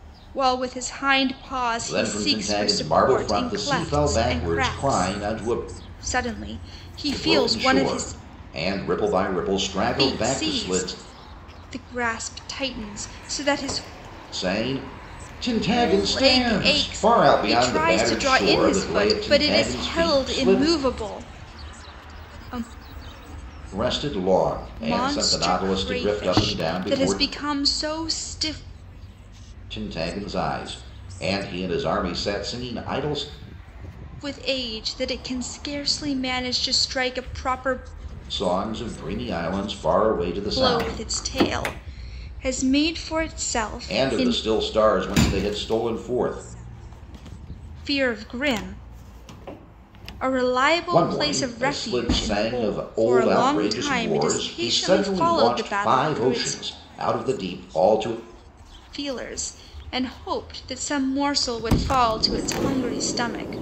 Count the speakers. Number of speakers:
2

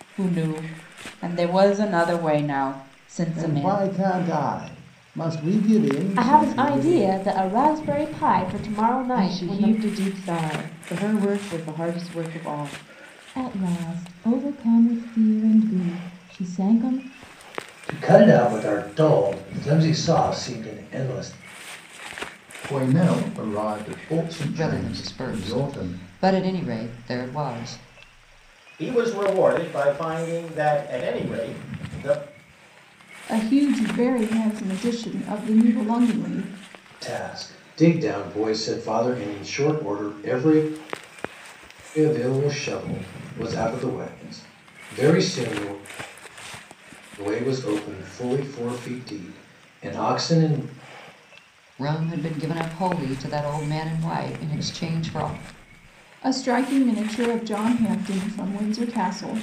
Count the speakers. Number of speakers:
10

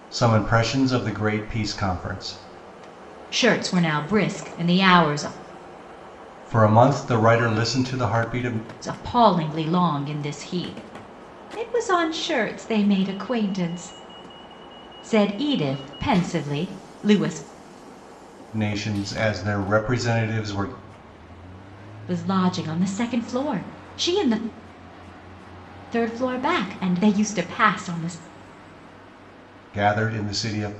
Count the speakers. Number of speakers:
2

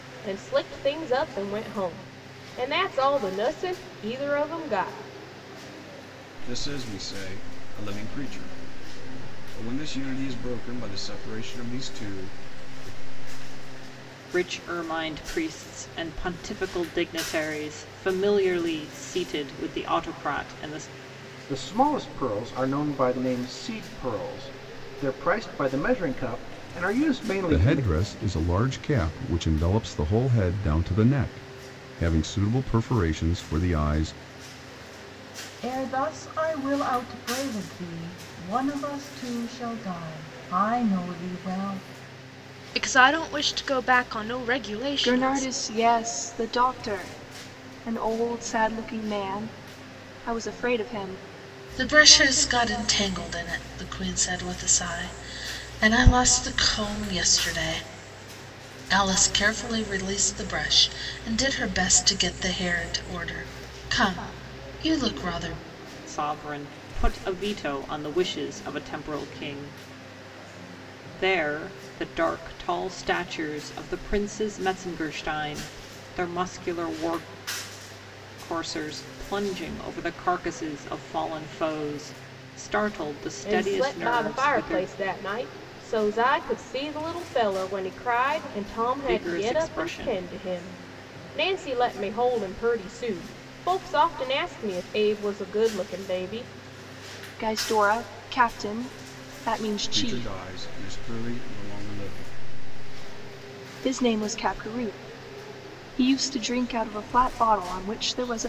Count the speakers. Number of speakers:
9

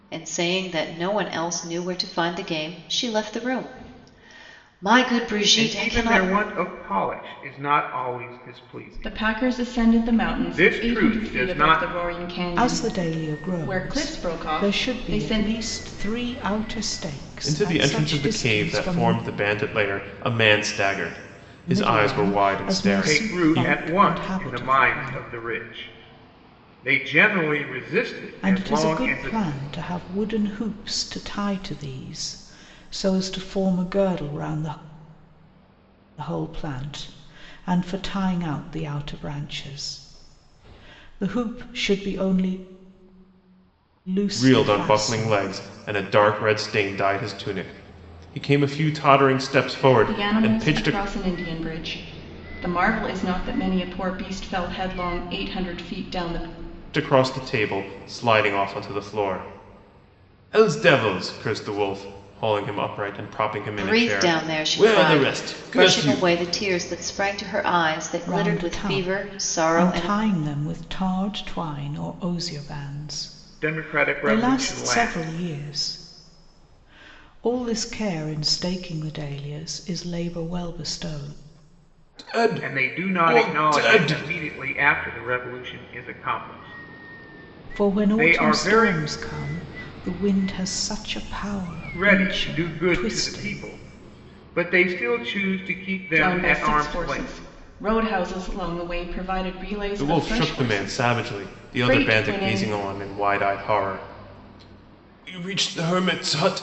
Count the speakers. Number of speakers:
5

